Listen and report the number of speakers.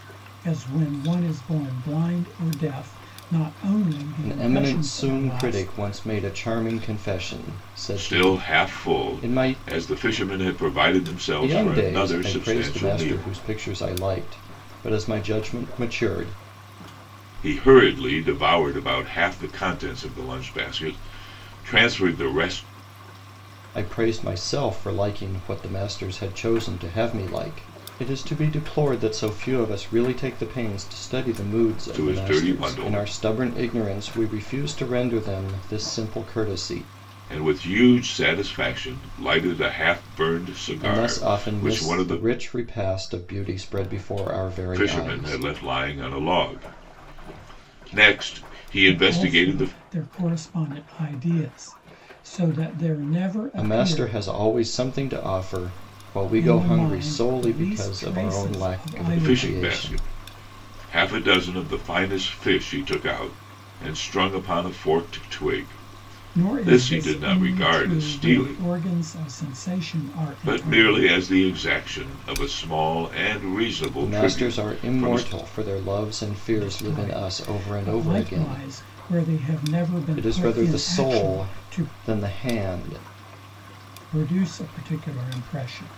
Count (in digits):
3